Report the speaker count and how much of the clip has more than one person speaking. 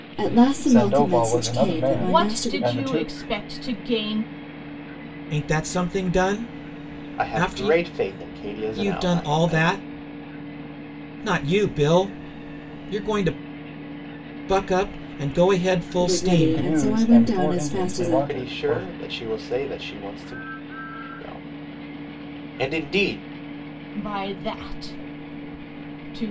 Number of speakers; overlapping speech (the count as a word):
five, about 26%